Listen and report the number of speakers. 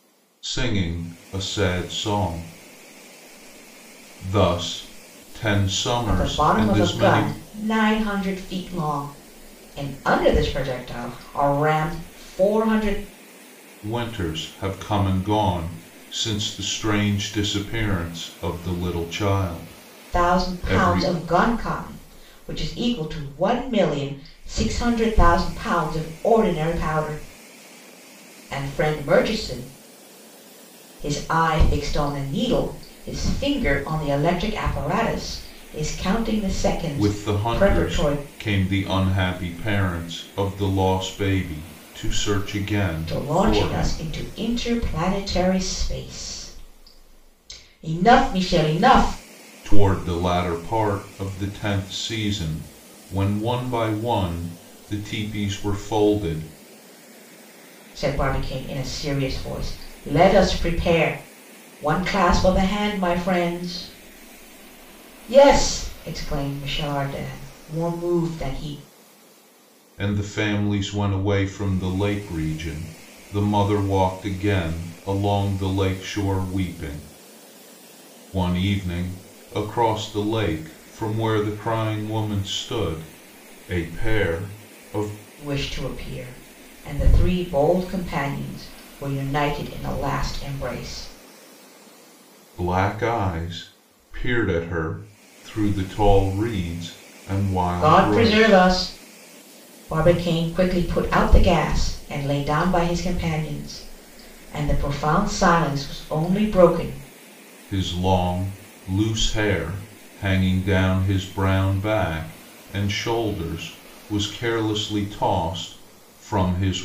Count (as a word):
two